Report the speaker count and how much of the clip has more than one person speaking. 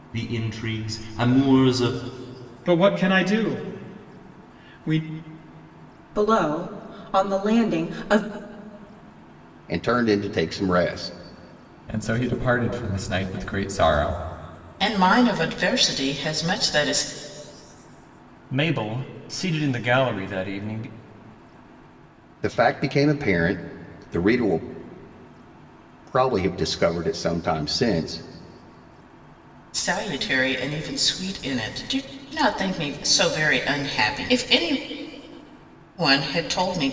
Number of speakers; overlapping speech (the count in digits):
7, no overlap